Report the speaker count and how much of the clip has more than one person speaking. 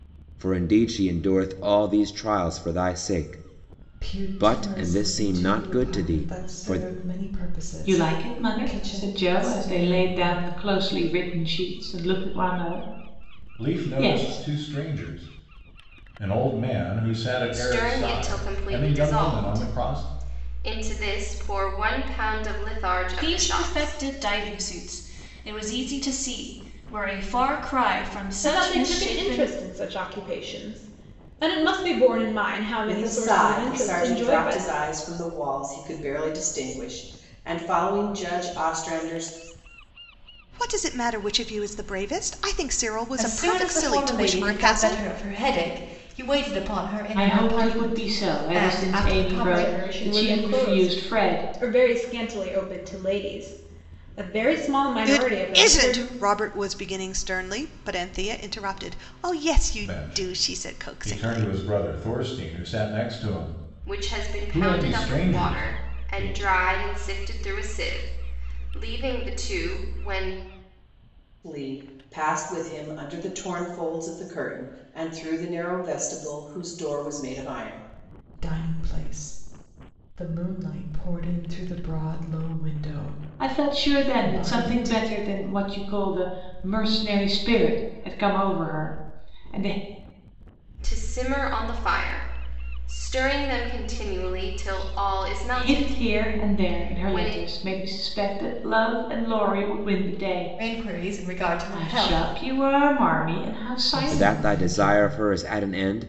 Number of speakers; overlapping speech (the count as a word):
ten, about 29%